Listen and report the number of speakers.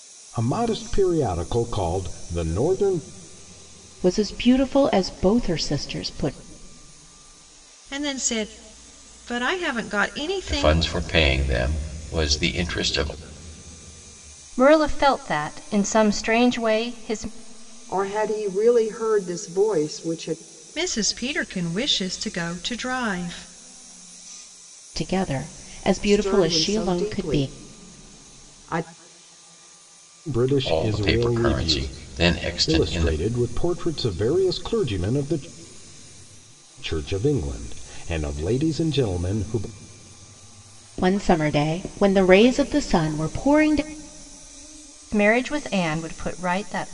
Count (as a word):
six